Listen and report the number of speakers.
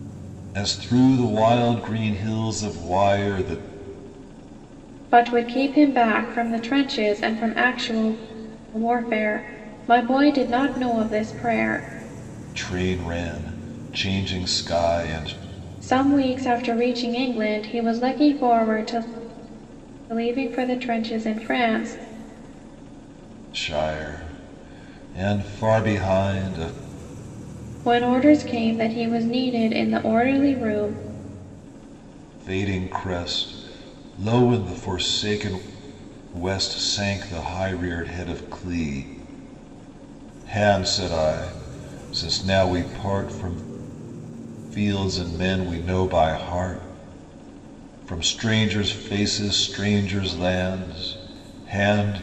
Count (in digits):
2